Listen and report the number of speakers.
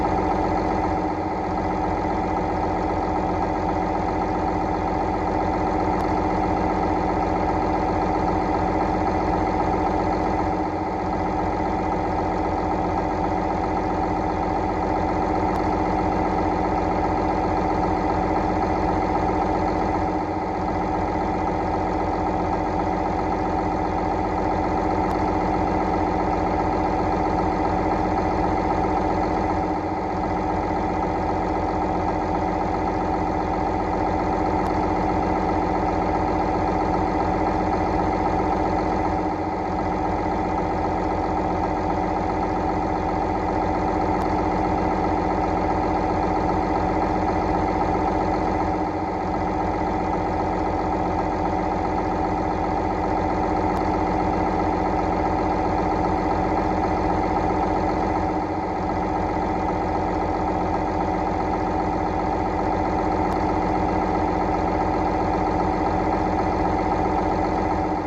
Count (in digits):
0